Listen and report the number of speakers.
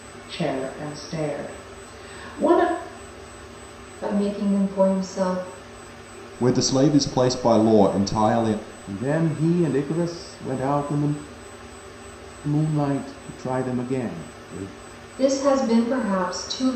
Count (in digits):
4